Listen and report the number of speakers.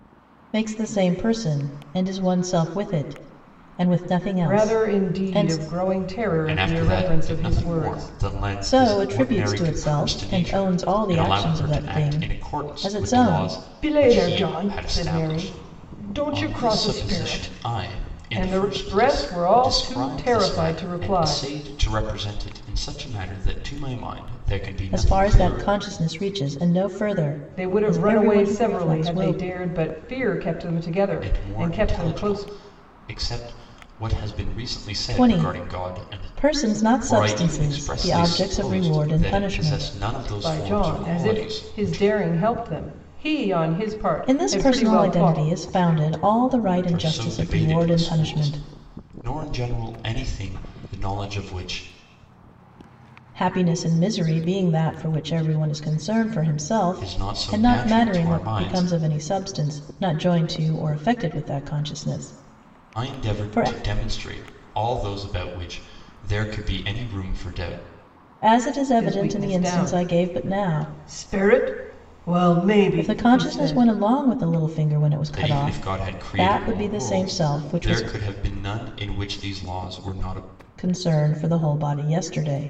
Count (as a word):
three